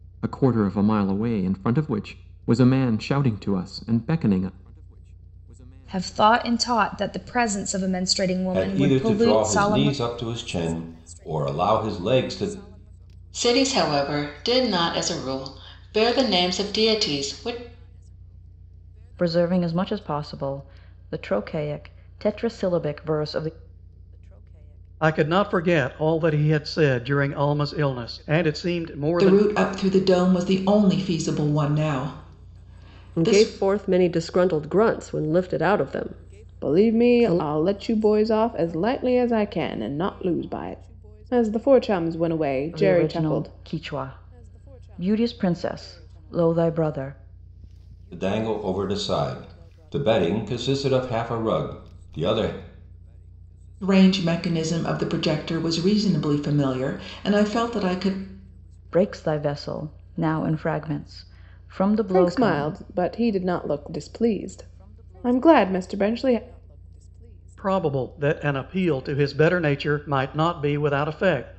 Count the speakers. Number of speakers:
9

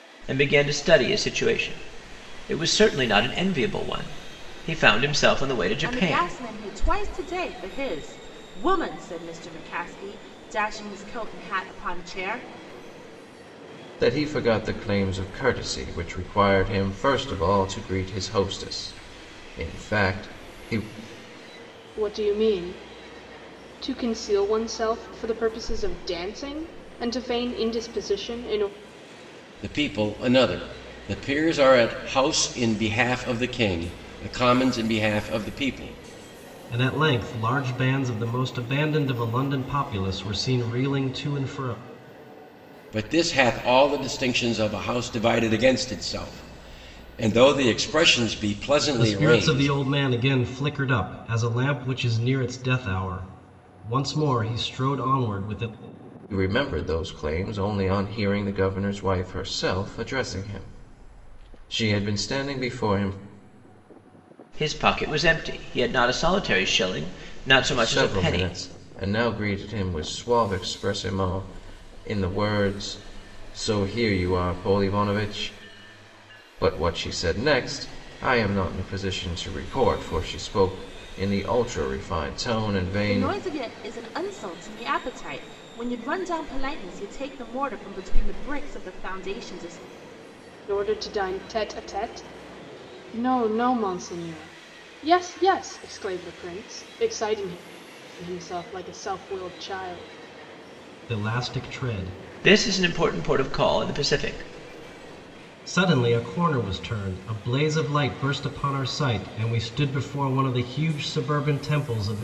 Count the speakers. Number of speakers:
6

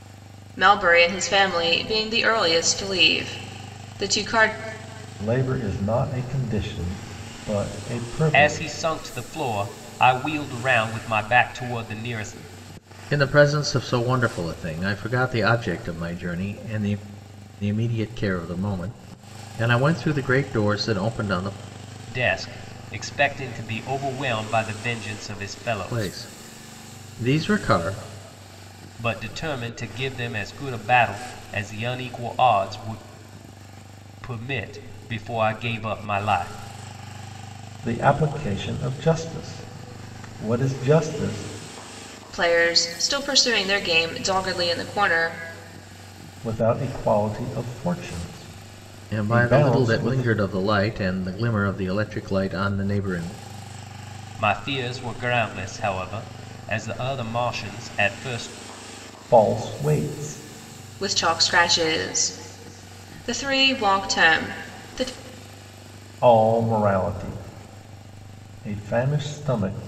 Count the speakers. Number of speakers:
4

